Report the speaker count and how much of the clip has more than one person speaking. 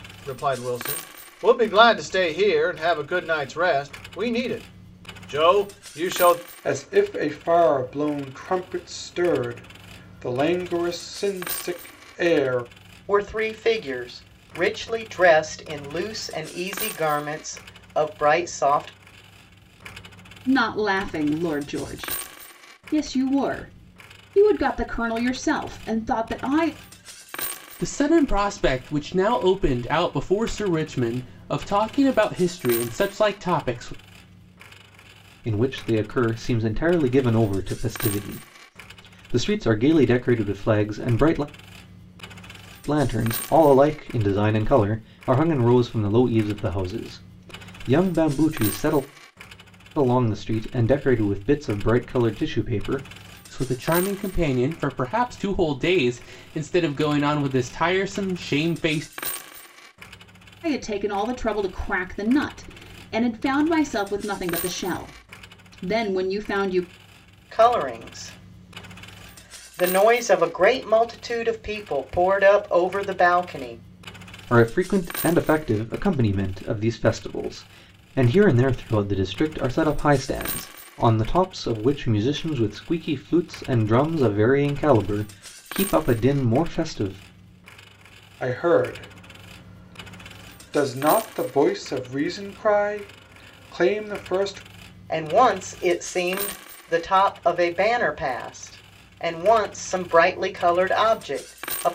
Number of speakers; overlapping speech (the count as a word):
six, no overlap